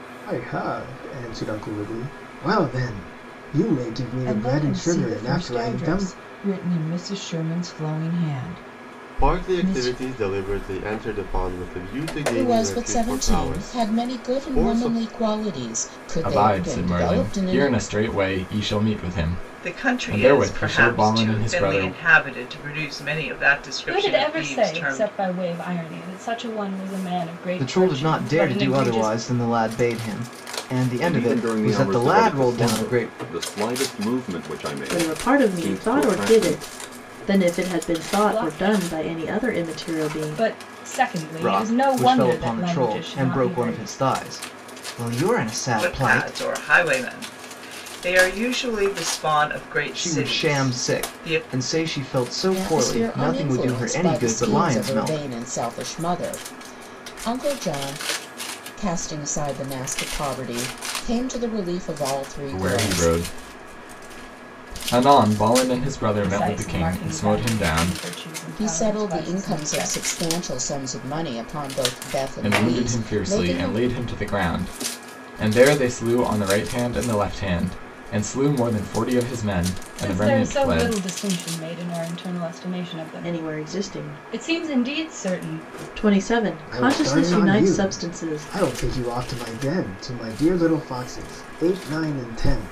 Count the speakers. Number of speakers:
ten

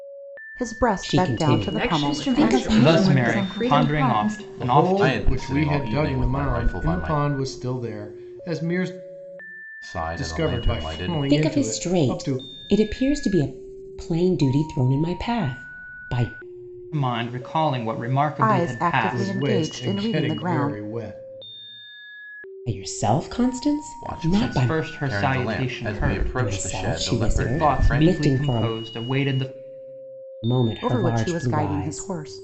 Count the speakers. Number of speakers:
seven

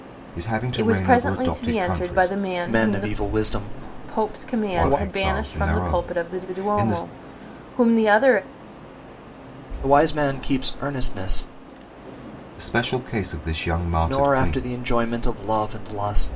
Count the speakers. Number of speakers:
three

